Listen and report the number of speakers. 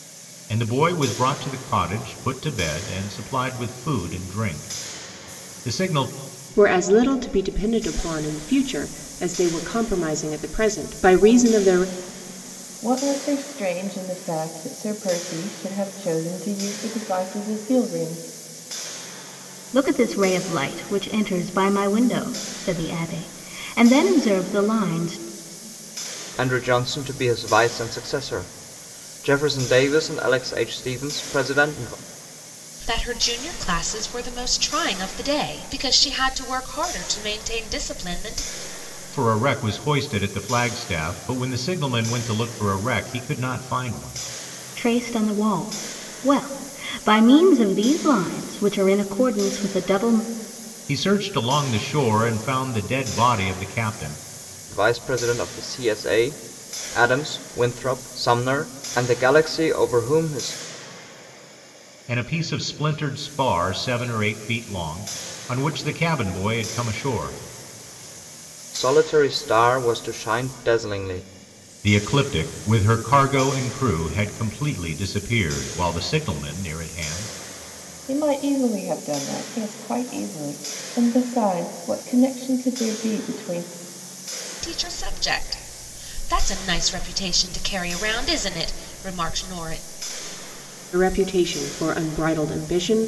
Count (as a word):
six